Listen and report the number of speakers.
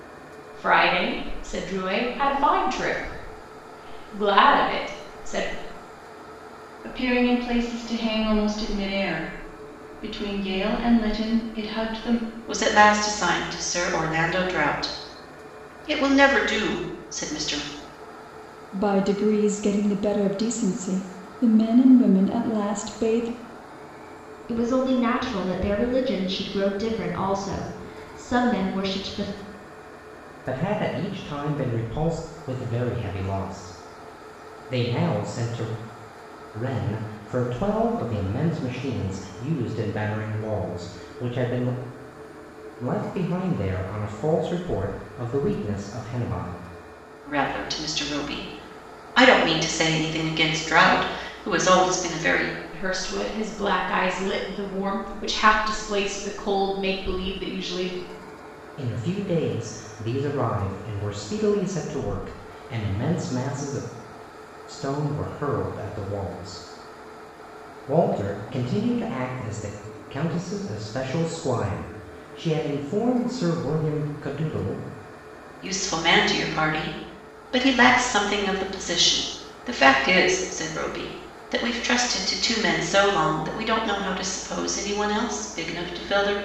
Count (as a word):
six